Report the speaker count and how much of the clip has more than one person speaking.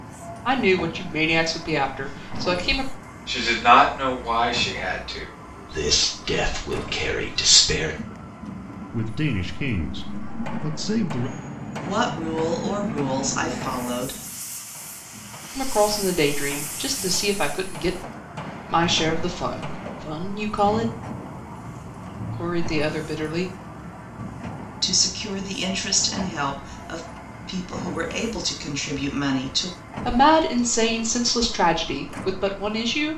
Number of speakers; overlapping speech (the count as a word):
five, no overlap